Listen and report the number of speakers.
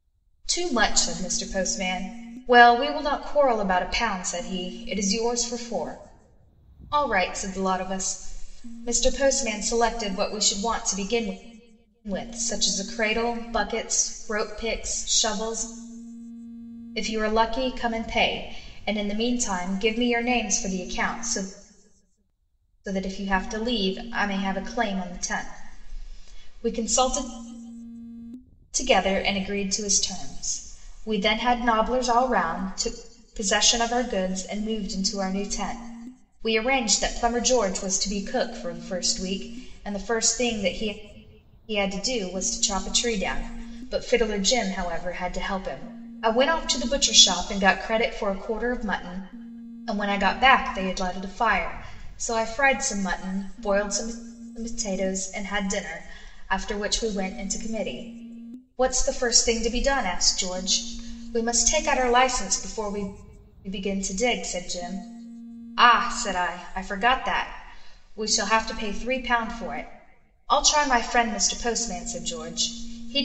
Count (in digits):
1